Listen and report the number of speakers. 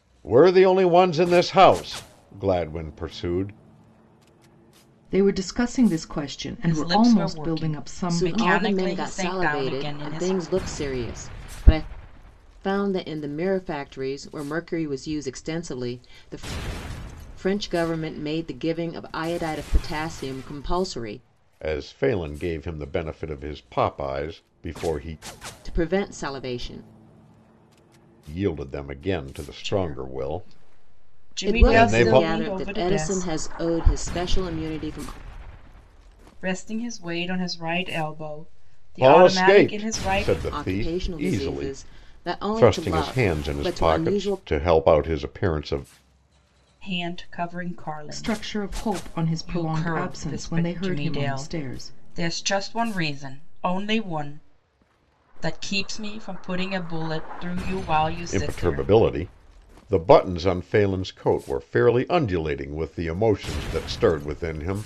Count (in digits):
4